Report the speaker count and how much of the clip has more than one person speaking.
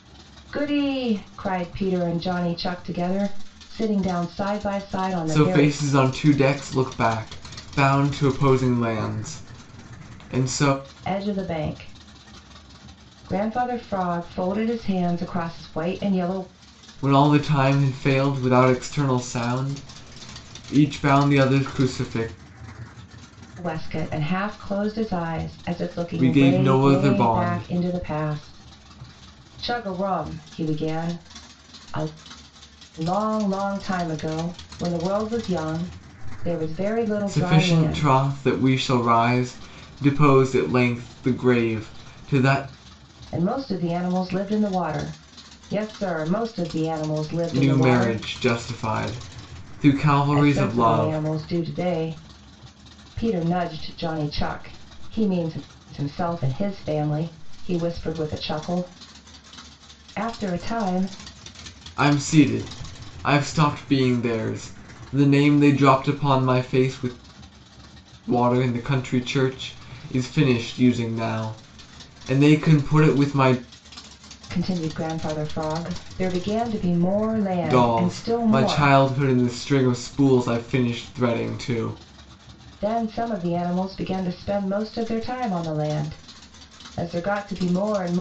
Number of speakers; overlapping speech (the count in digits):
2, about 7%